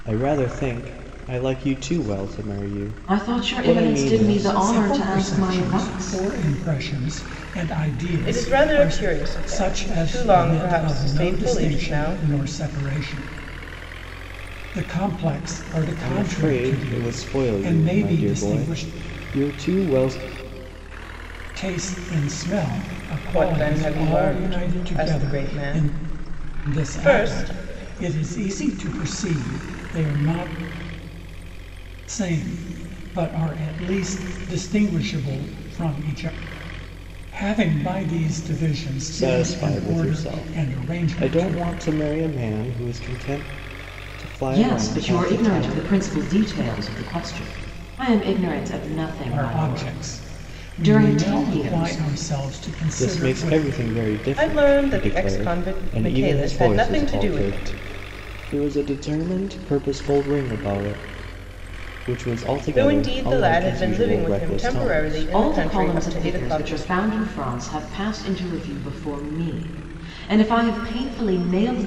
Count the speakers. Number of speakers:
four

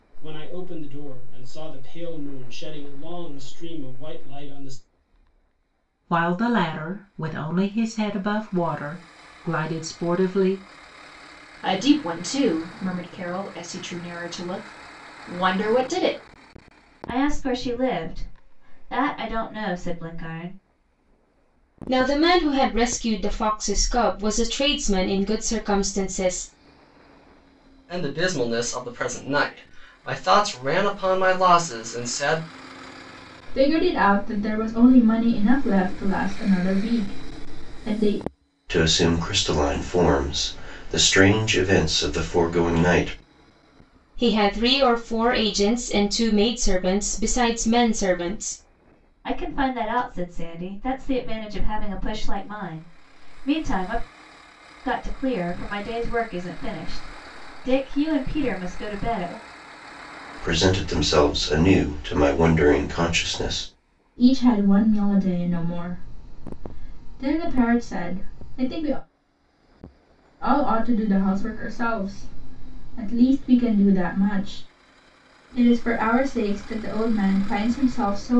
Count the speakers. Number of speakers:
eight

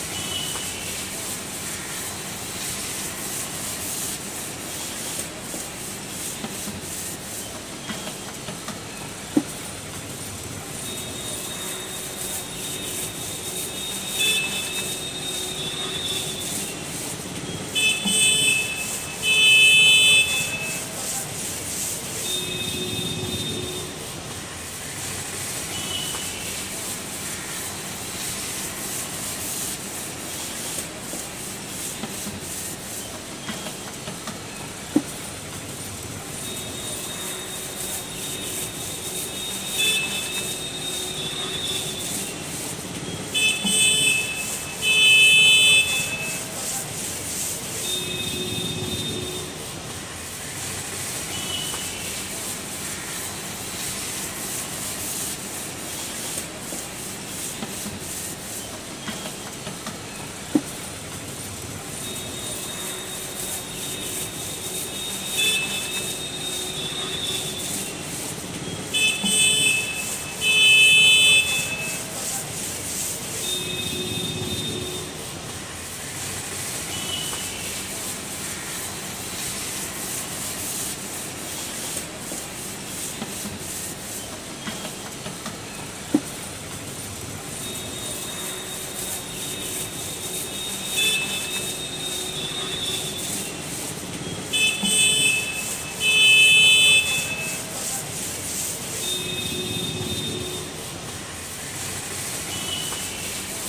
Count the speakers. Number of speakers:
zero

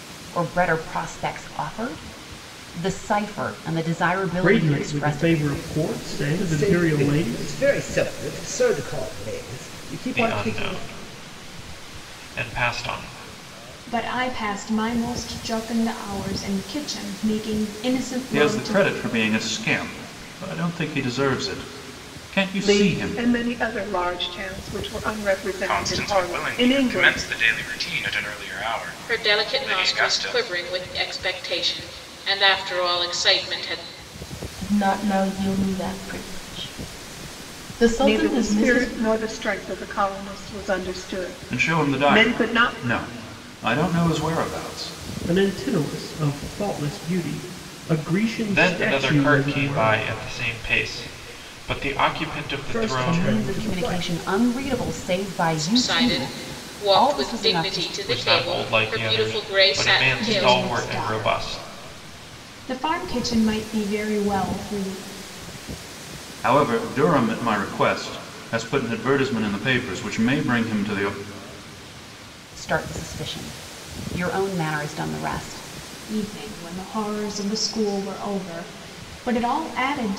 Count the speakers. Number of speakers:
ten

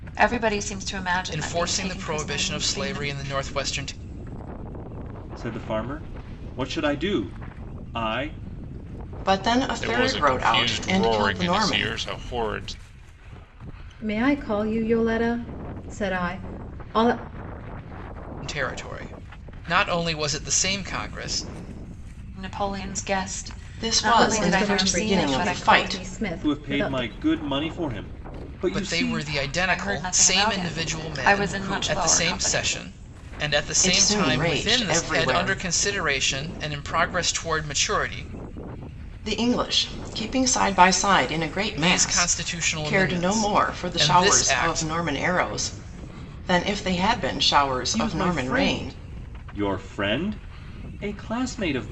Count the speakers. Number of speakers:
six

